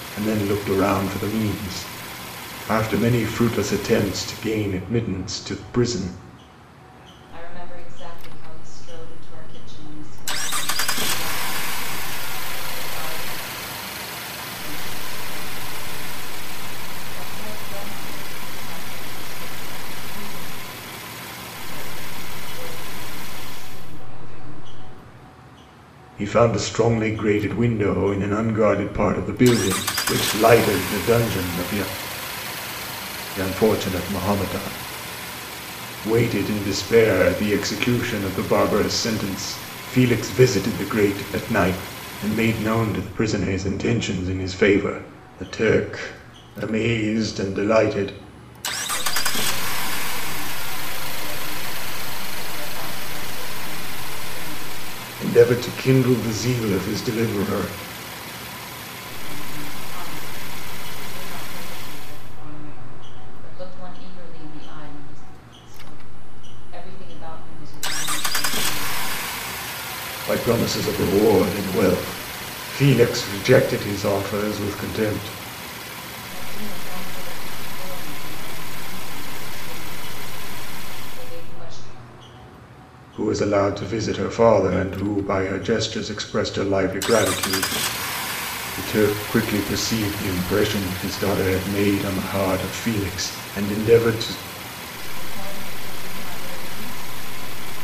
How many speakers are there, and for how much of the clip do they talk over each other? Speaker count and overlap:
two, no overlap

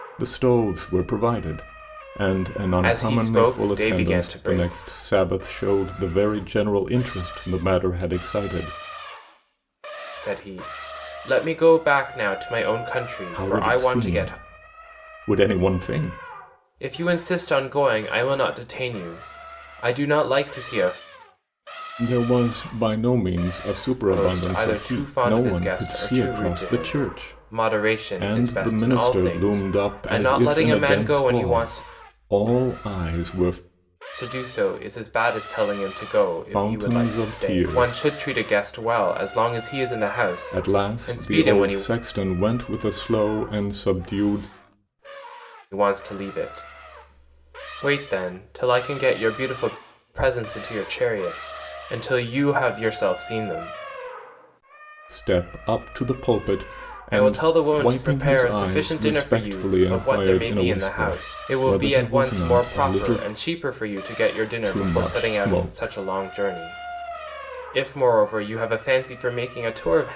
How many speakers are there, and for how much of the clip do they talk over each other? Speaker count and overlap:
two, about 30%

